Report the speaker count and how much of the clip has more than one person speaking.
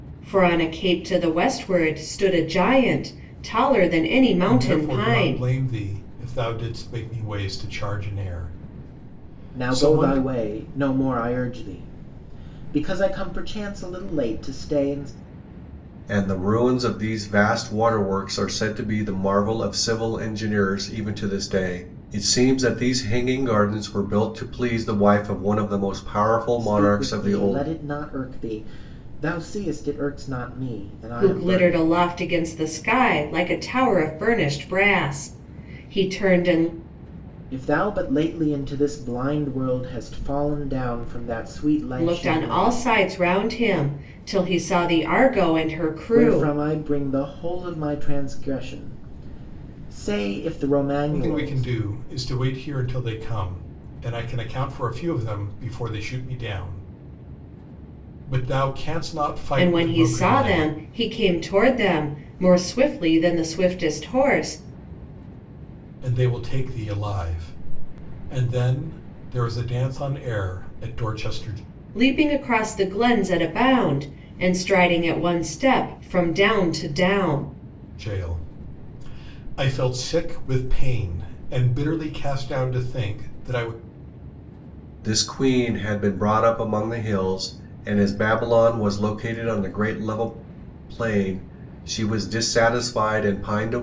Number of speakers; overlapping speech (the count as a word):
four, about 7%